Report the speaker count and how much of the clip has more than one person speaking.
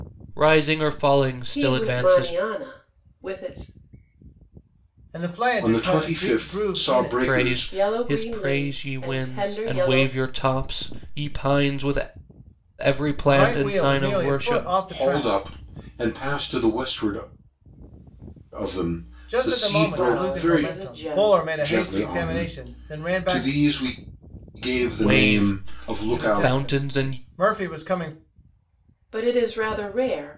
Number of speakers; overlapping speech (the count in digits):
4, about 46%